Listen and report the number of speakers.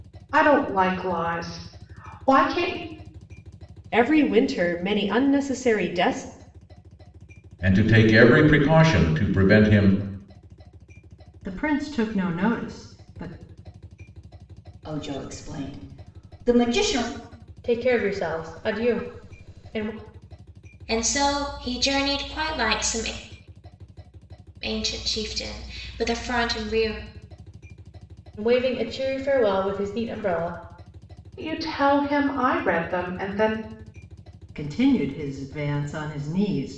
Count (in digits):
7